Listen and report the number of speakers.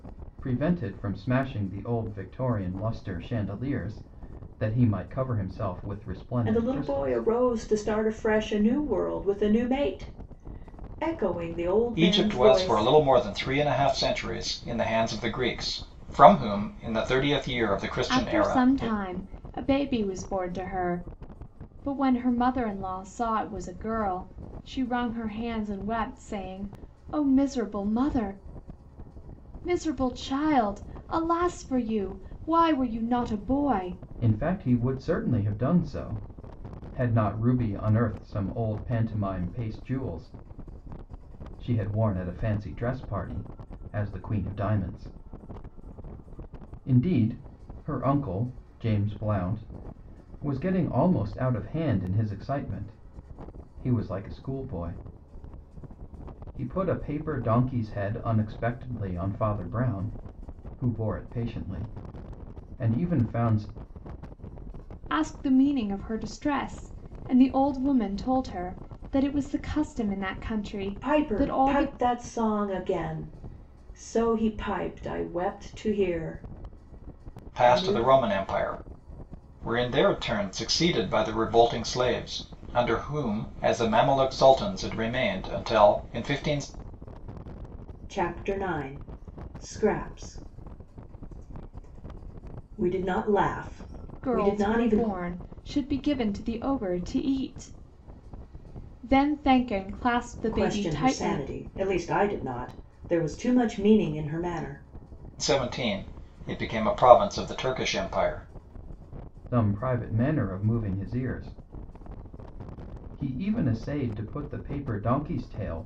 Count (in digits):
4